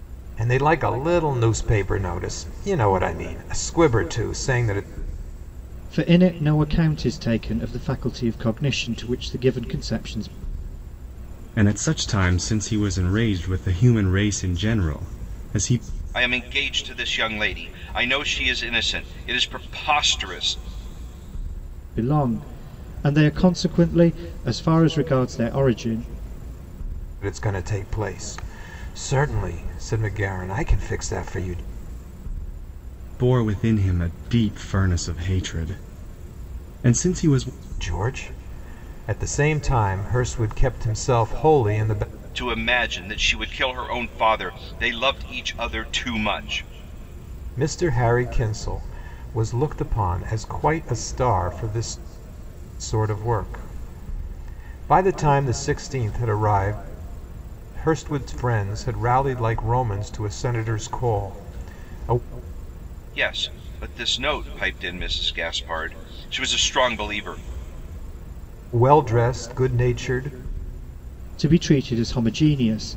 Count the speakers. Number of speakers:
4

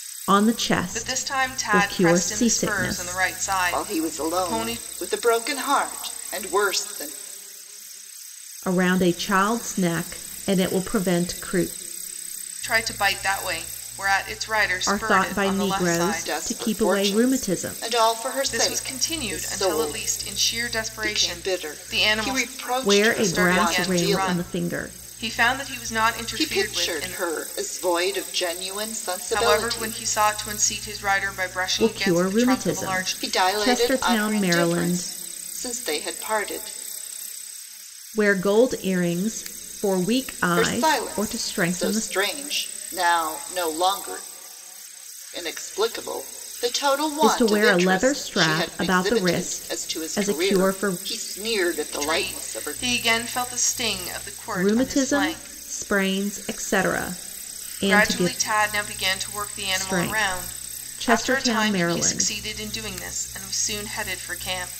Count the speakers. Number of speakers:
3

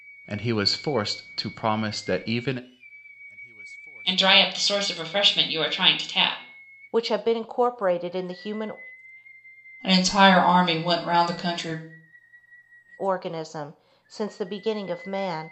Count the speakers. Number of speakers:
4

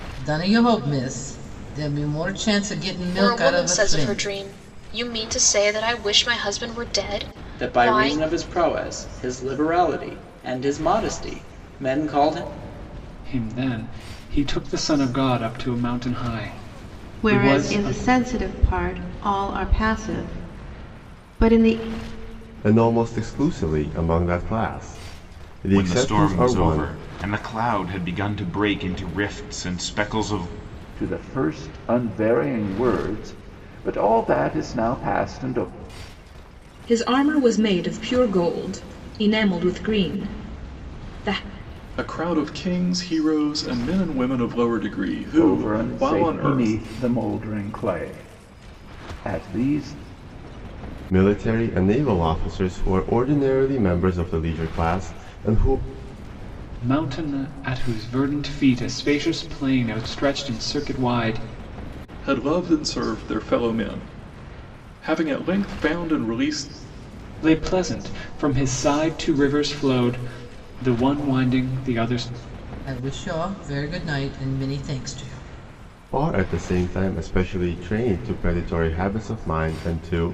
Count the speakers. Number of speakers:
10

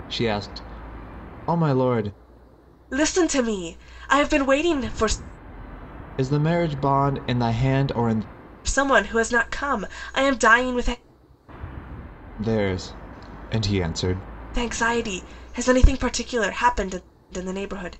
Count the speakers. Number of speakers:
2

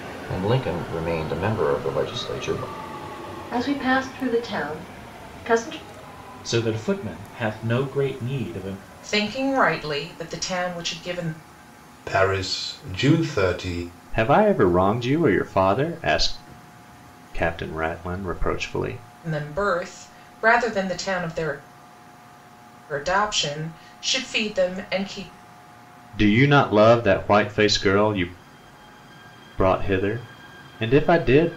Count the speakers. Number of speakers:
6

